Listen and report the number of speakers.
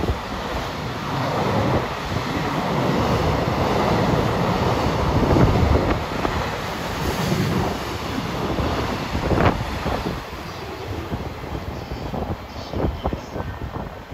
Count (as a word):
zero